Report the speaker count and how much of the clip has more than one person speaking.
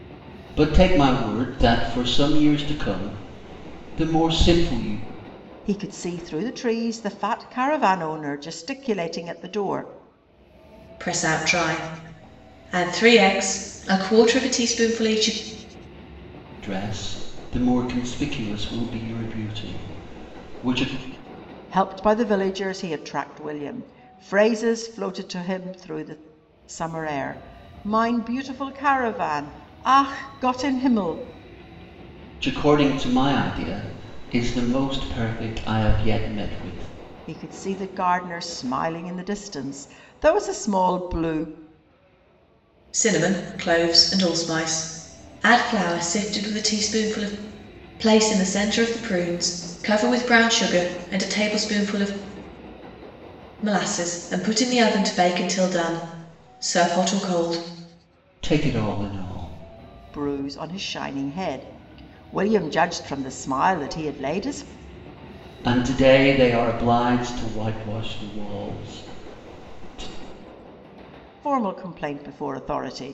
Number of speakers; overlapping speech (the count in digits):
3, no overlap